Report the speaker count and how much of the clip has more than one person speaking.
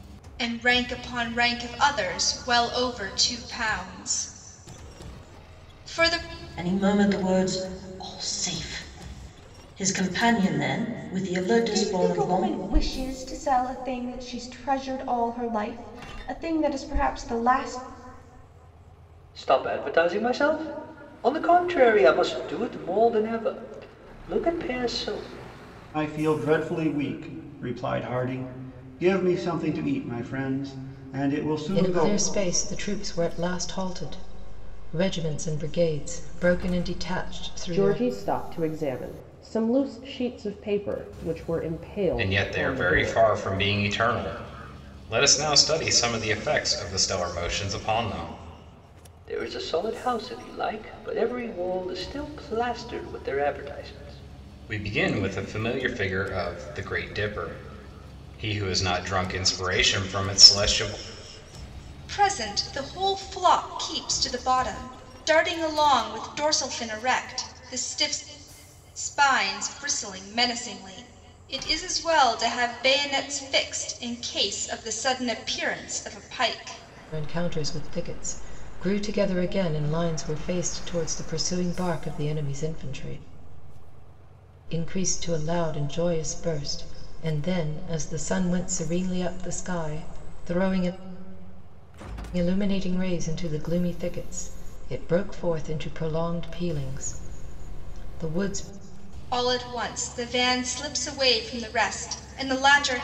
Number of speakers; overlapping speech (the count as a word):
eight, about 3%